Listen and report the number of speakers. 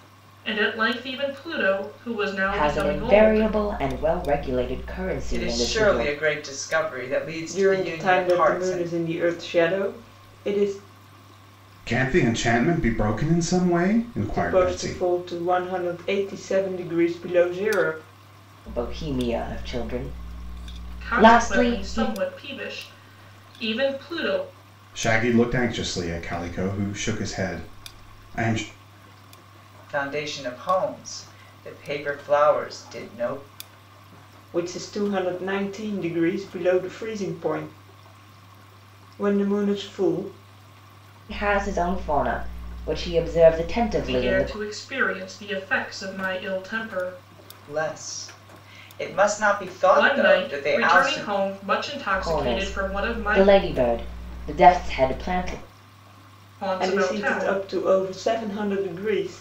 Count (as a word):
five